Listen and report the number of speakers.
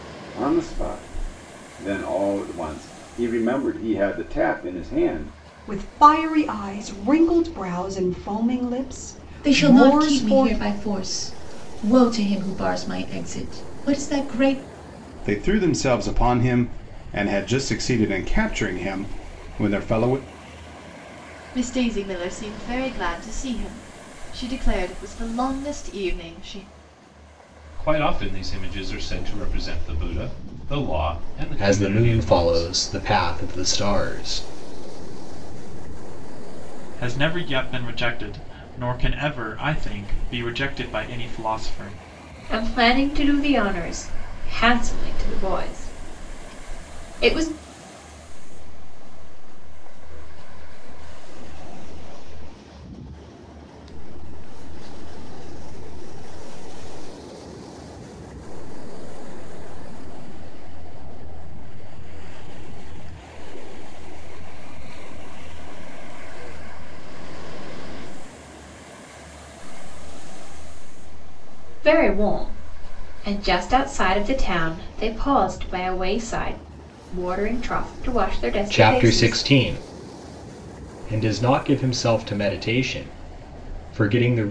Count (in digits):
10